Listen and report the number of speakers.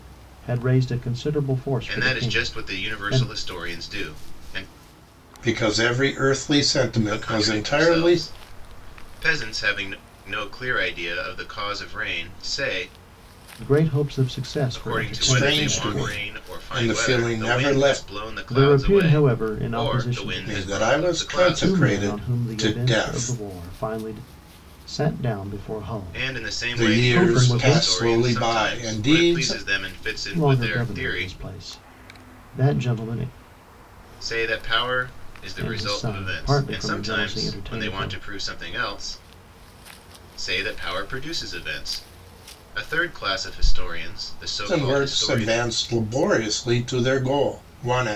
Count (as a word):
three